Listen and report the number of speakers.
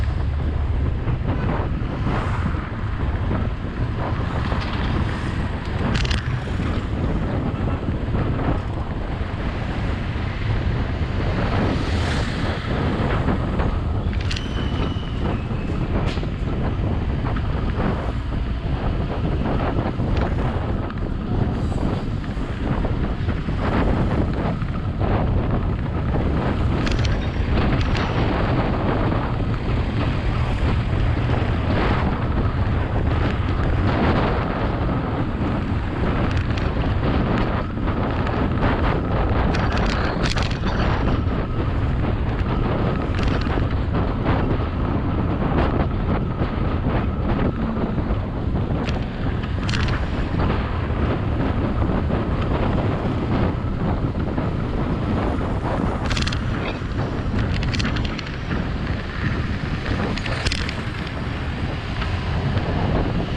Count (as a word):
zero